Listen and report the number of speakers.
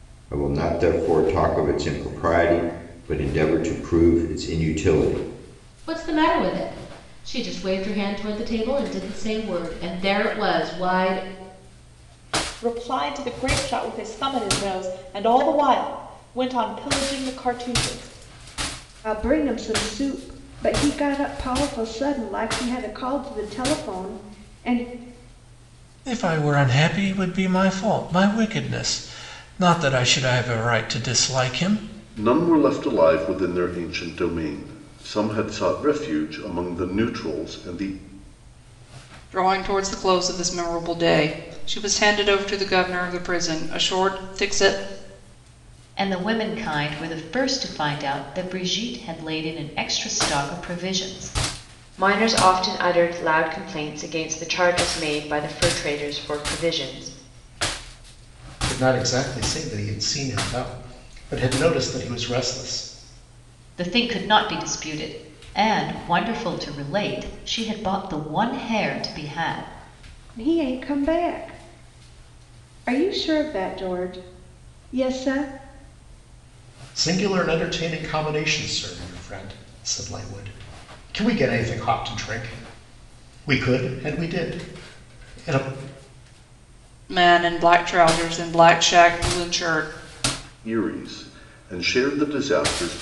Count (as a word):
ten